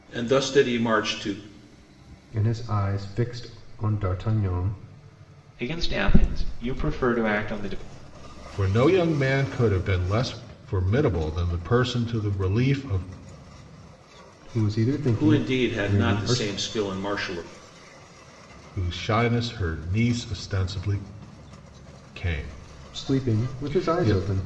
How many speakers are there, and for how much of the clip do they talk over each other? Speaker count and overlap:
4, about 11%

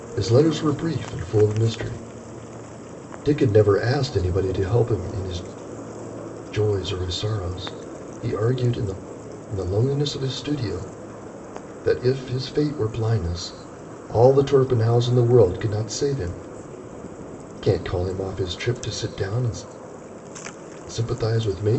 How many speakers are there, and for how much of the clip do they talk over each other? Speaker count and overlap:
1, no overlap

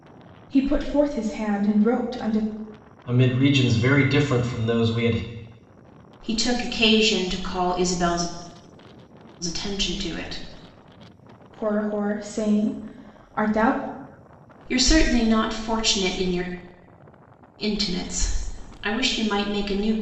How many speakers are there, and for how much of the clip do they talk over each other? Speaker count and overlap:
3, no overlap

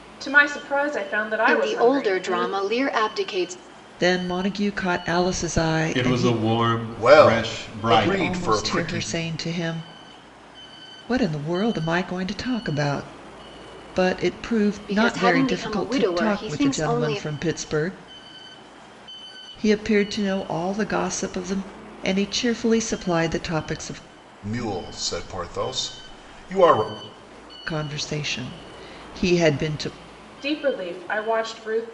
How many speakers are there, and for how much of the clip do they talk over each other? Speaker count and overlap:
5, about 19%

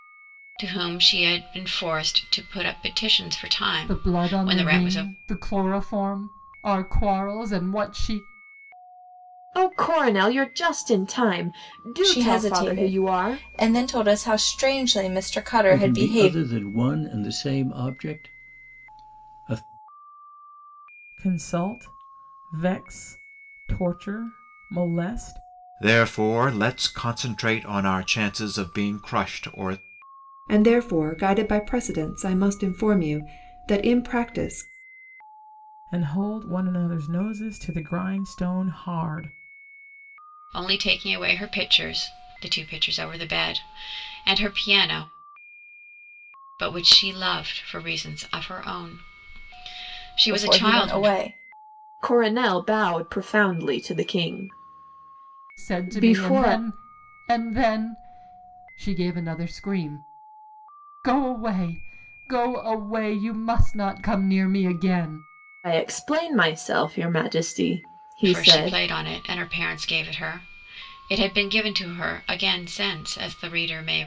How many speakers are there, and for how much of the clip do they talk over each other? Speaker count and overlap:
8, about 8%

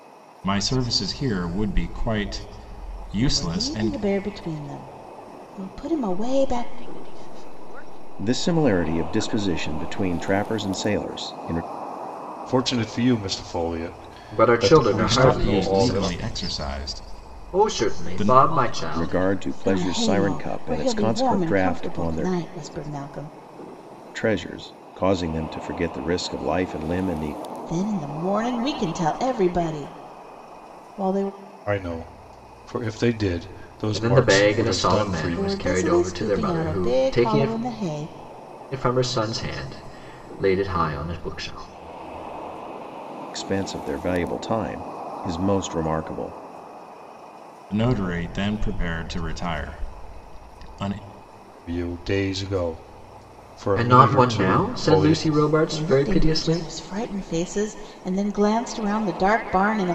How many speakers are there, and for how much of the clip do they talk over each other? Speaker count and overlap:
6, about 27%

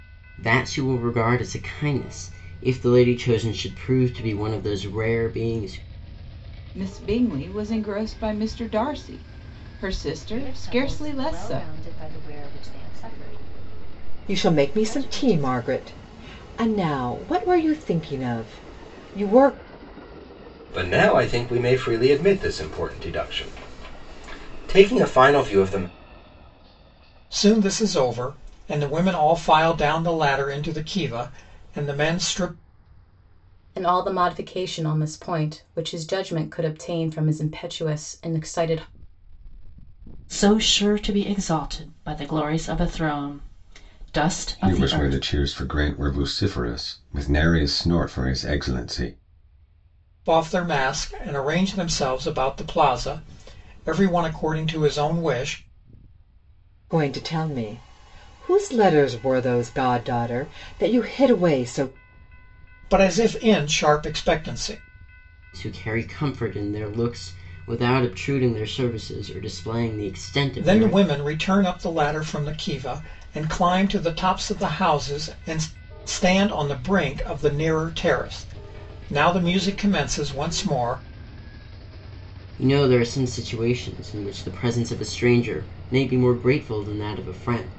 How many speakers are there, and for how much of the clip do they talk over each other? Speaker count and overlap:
9, about 4%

